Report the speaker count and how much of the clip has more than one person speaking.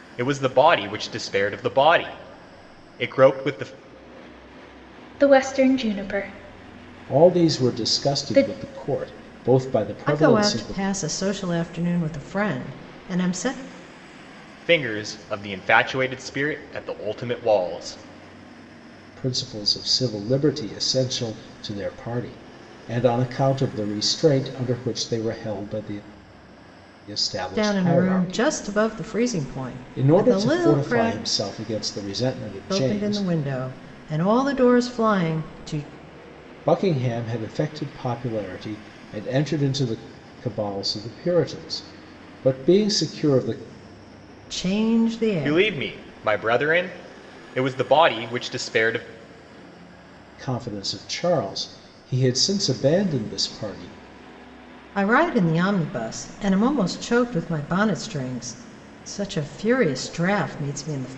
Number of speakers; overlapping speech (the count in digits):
4, about 9%